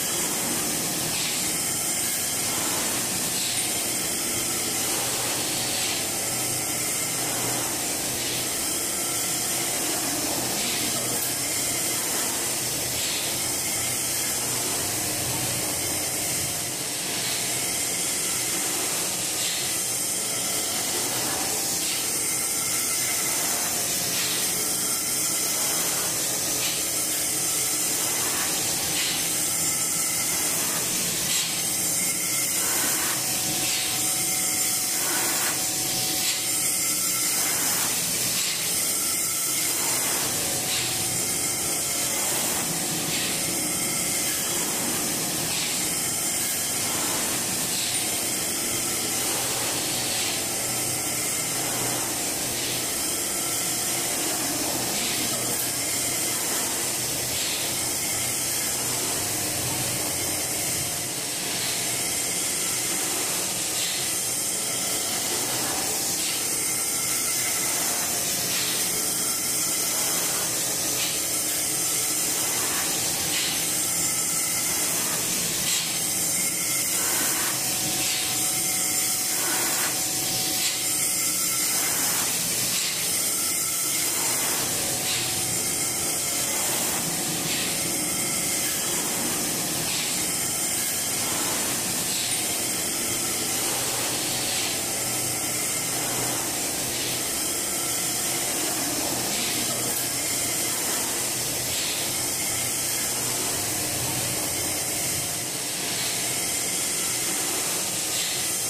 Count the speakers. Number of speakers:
0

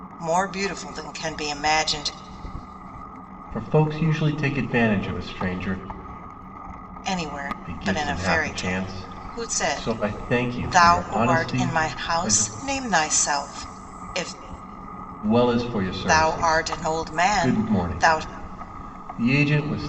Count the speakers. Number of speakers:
2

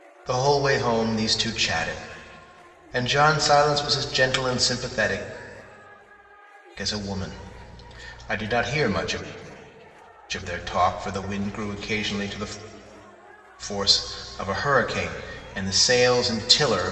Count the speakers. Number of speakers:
1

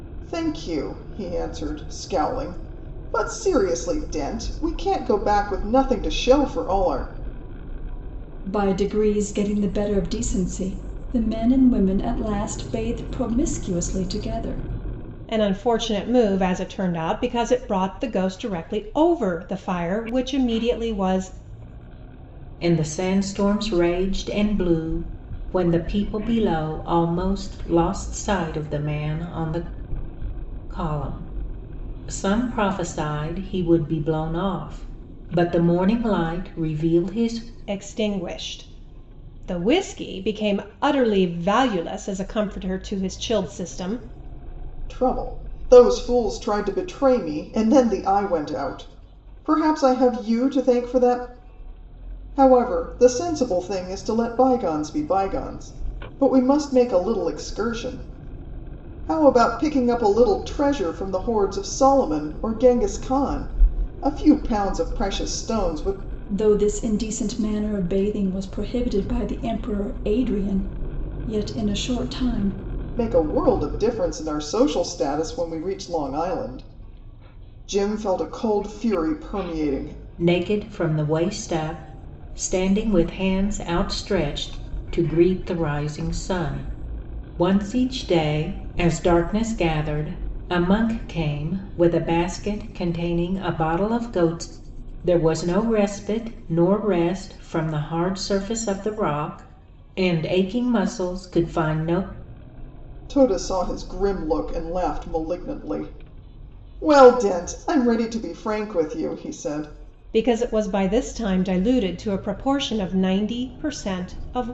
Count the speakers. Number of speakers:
4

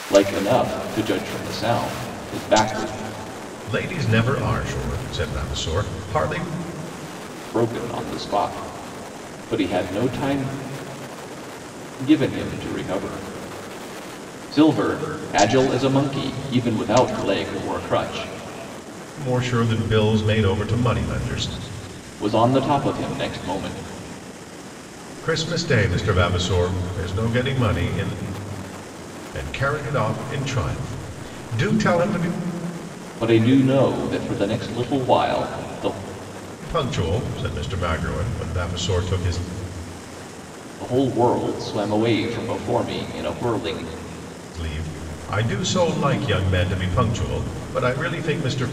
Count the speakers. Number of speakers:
2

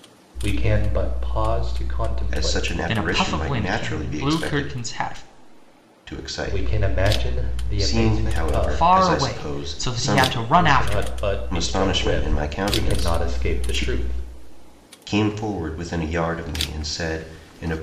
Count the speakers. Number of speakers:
3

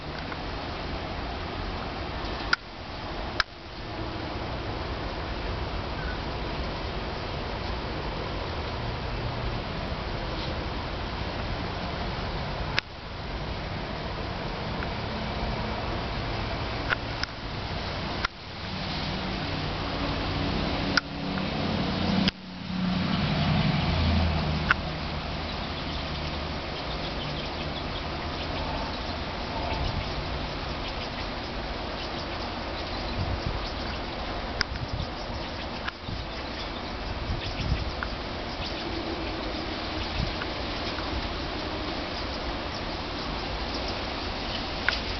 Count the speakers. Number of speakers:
0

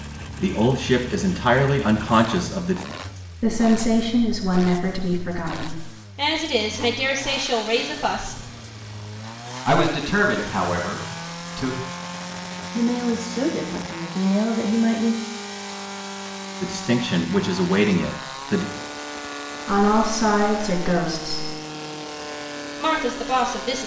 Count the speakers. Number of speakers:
5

